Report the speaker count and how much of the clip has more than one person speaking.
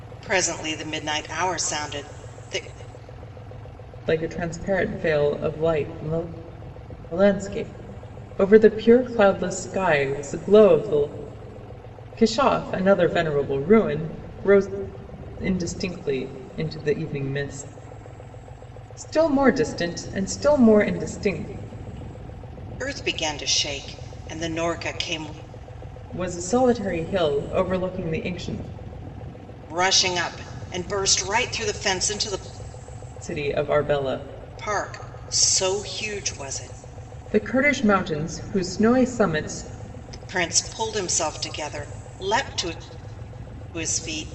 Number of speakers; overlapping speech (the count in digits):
2, no overlap